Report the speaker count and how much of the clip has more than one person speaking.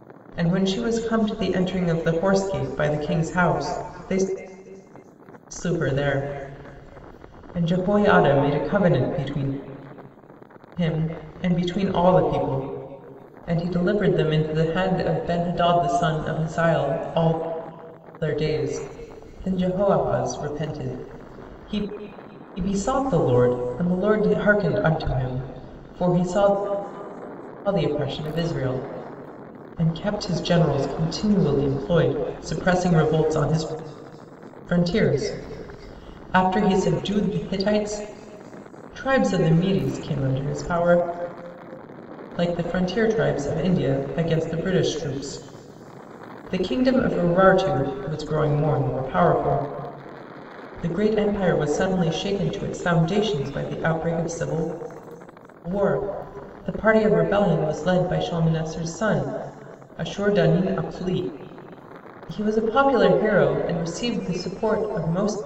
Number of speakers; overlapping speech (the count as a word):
one, no overlap